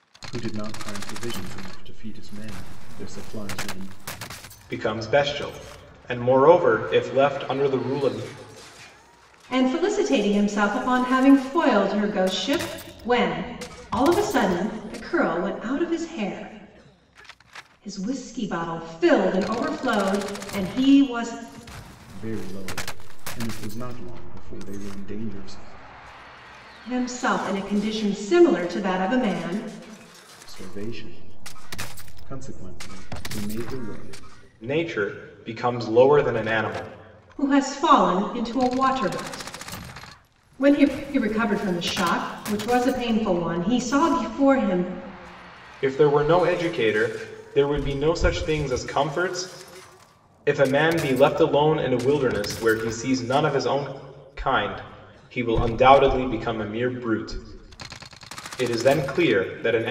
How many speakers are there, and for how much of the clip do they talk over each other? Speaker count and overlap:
three, no overlap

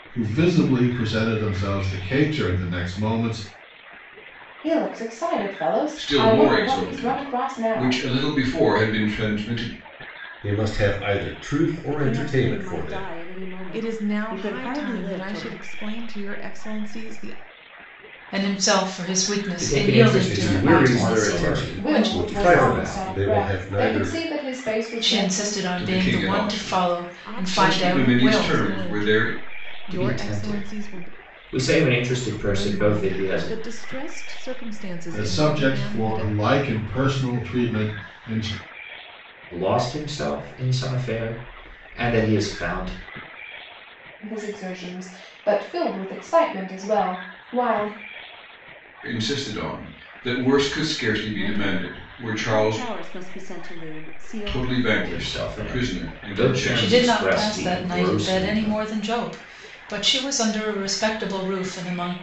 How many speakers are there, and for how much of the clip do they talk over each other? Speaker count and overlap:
eight, about 38%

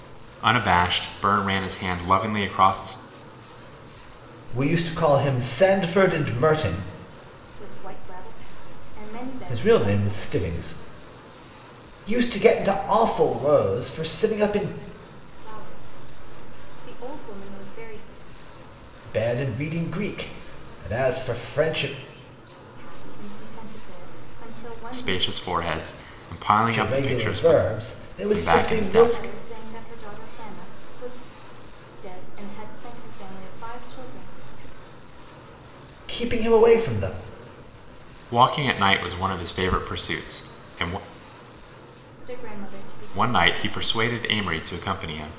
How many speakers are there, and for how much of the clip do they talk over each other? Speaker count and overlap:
three, about 9%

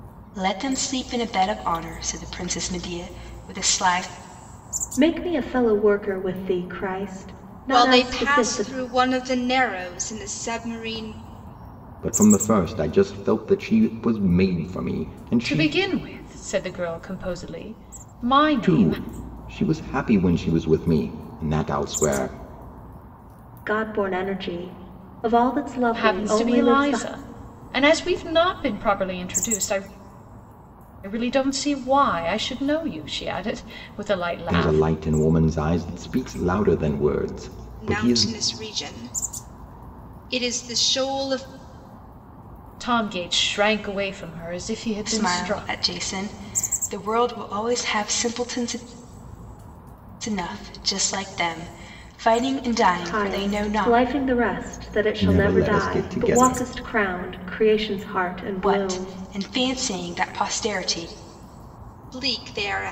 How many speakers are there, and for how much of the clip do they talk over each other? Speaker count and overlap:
five, about 12%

